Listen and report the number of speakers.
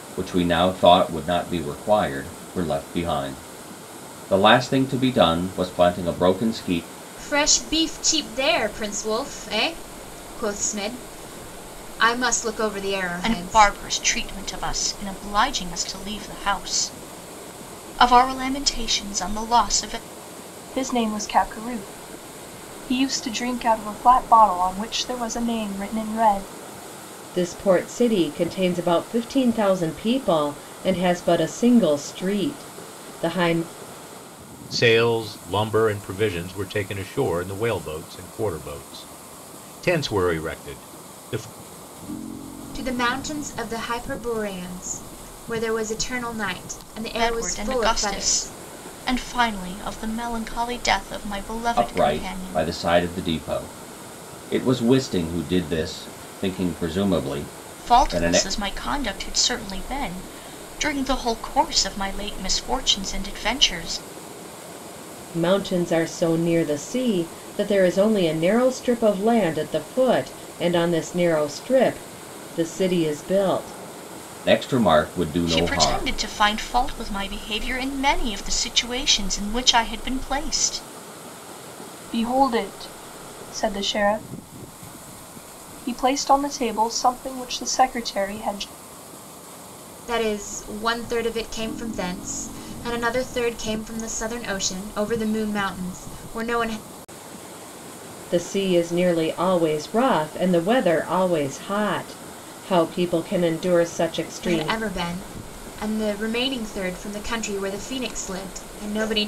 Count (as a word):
six